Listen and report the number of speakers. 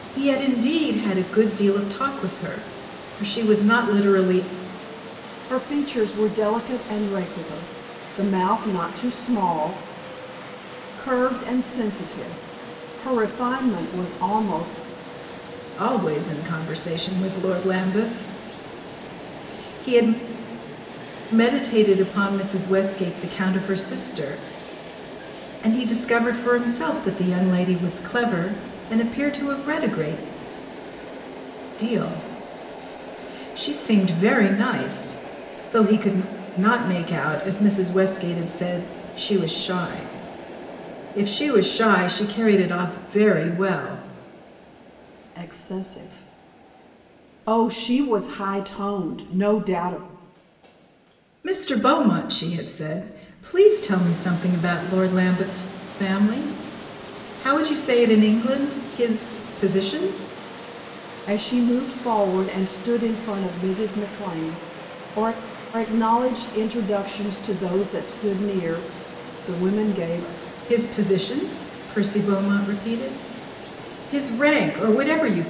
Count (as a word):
two